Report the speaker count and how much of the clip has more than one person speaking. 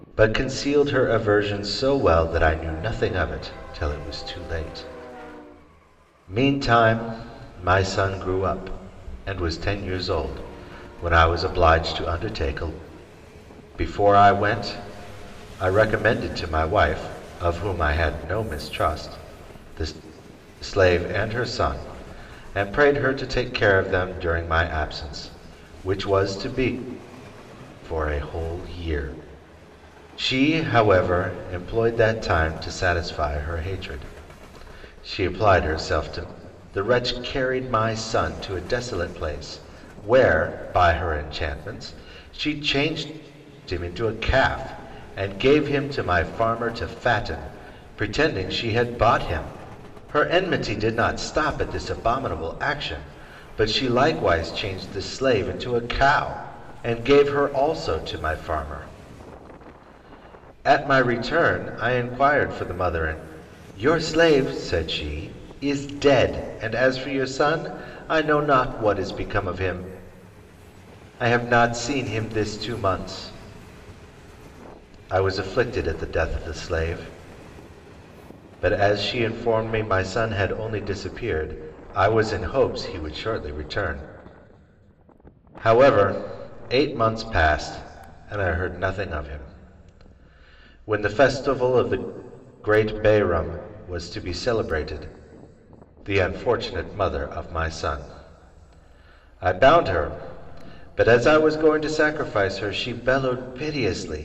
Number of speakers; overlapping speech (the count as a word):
one, no overlap